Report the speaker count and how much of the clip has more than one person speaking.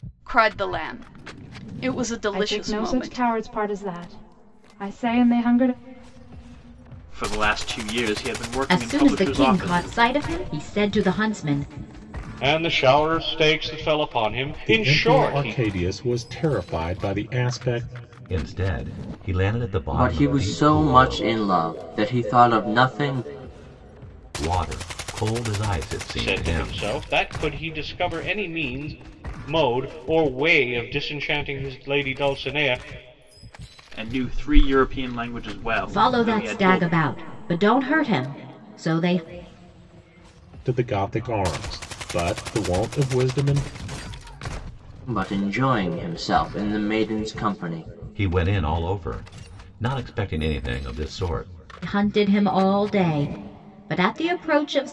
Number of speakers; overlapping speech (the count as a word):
eight, about 12%